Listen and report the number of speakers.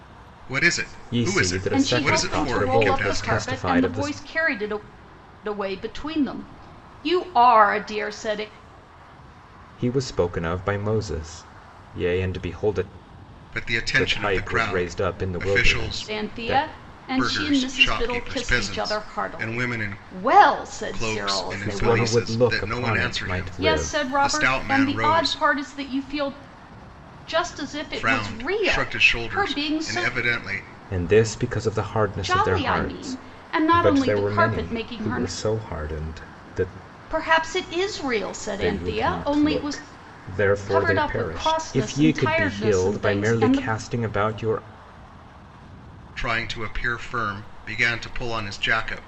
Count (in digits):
3